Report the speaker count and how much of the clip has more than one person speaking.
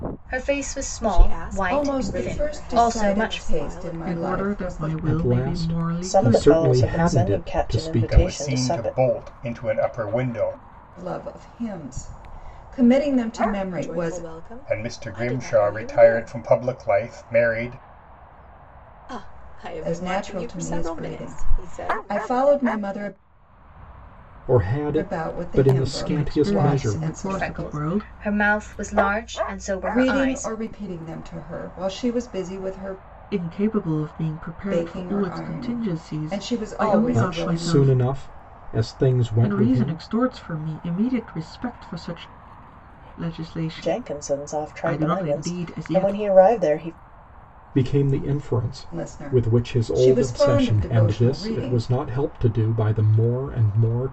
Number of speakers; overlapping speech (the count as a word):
seven, about 47%